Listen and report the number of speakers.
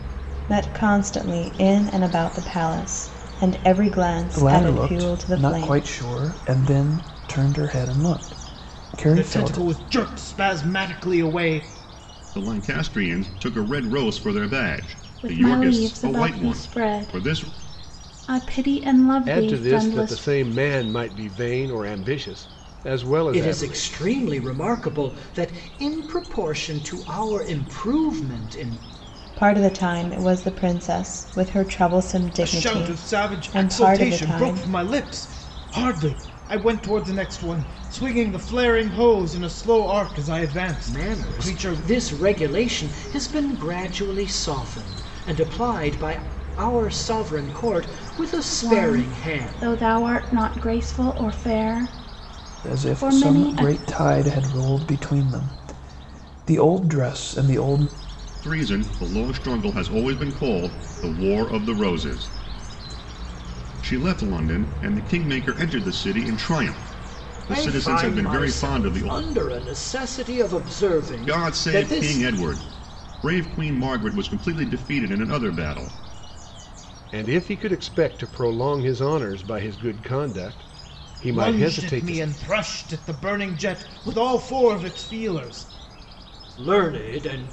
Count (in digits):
7